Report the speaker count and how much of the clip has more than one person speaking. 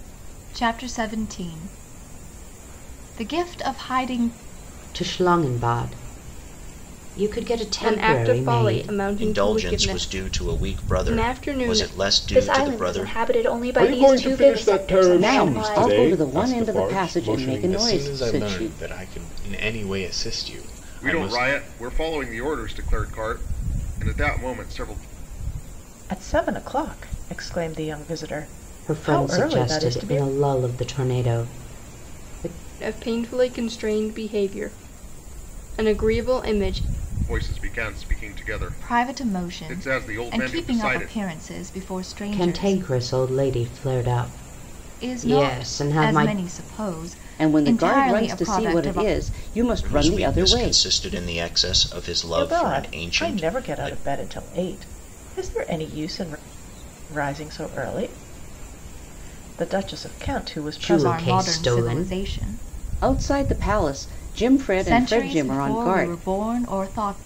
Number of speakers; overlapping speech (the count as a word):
ten, about 34%